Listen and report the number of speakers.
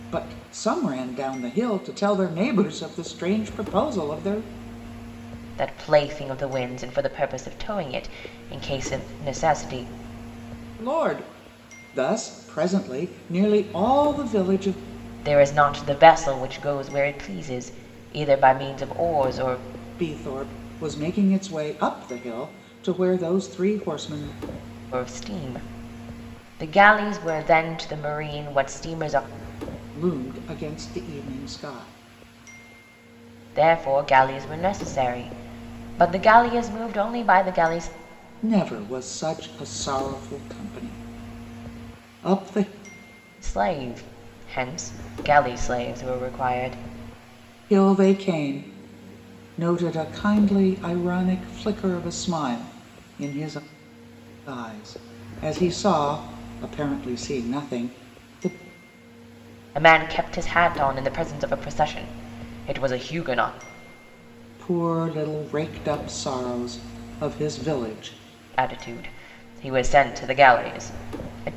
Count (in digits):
2